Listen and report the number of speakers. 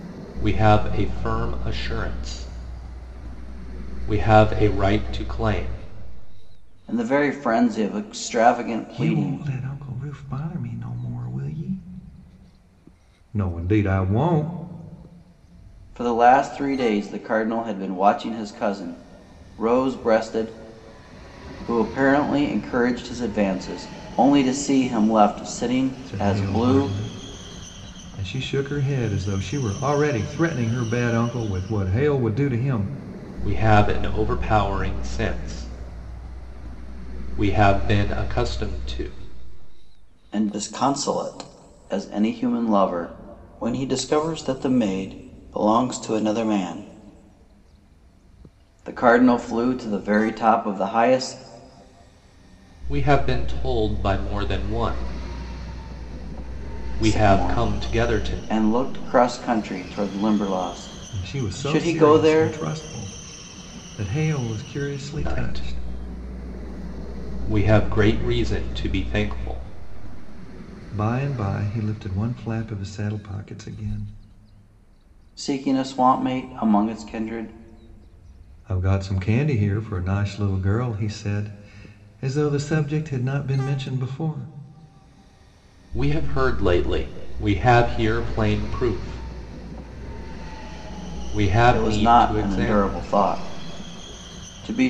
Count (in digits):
3